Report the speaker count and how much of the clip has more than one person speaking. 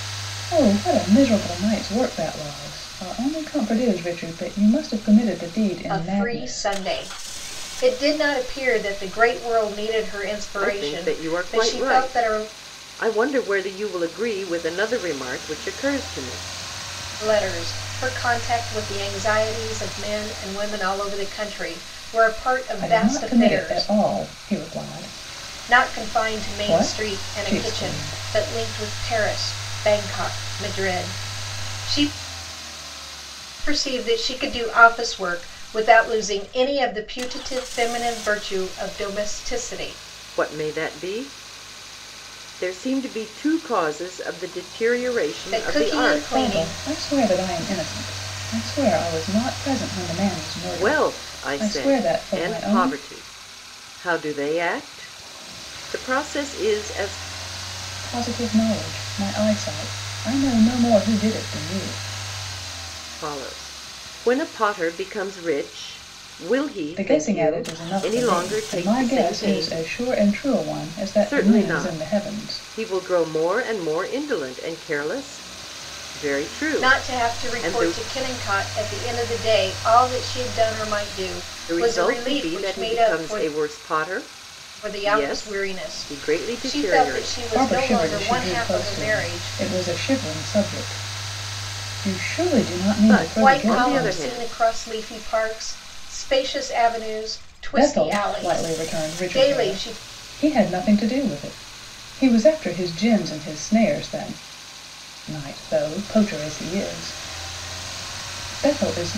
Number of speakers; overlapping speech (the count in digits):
3, about 24%